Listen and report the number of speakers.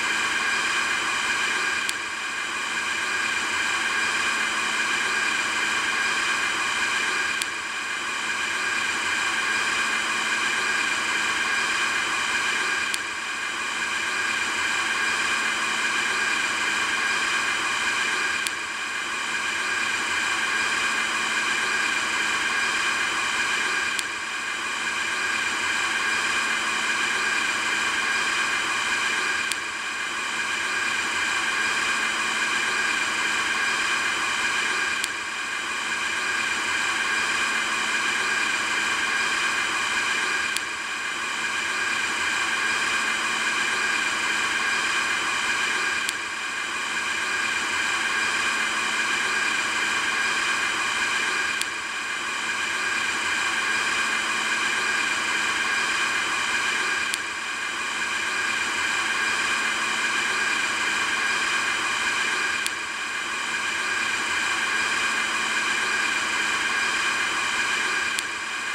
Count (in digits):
0